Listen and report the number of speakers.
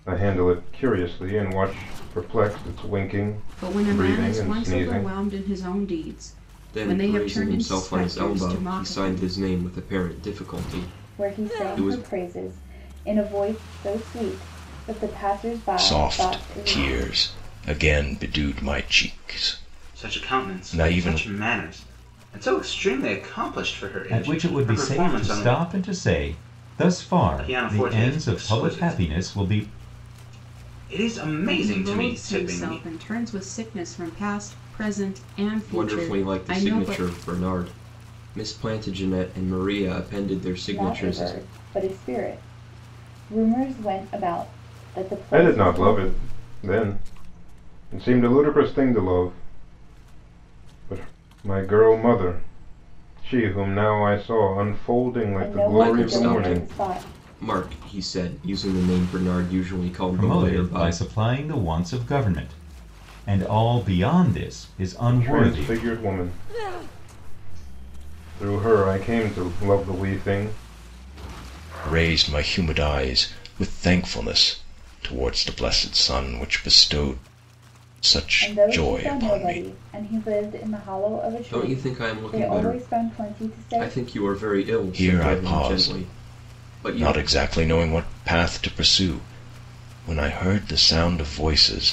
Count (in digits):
7